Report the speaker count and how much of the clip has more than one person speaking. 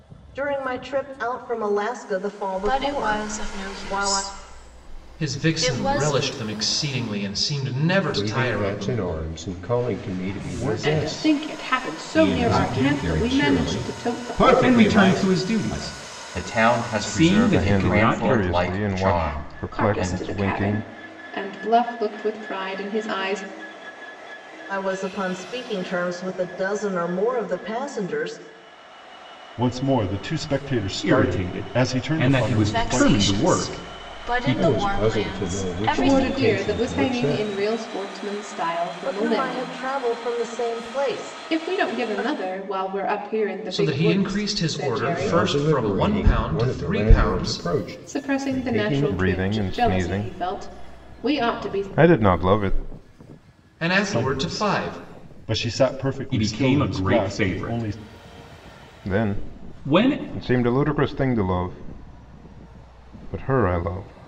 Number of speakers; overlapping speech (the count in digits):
10, about 52%